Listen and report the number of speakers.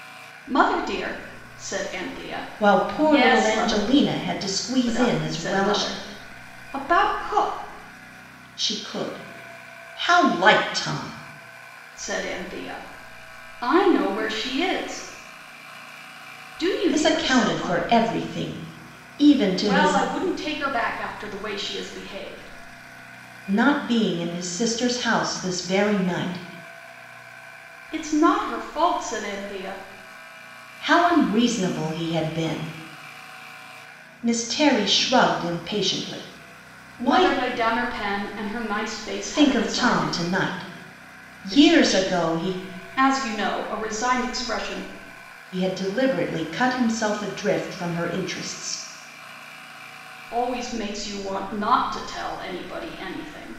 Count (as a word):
two